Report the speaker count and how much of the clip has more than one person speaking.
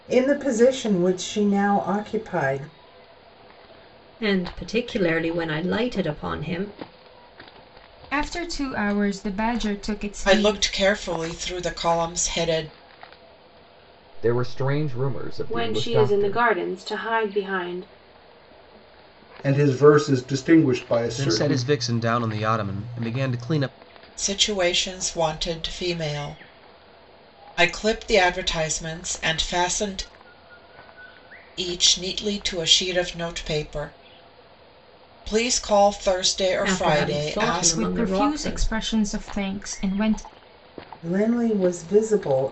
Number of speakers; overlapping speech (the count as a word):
eight, about 9%